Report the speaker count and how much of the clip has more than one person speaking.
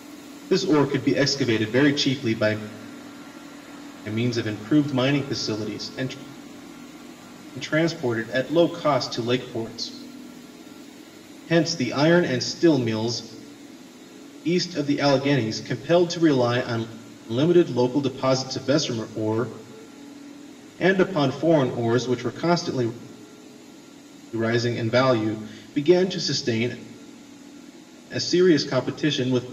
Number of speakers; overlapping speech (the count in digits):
1, no overlap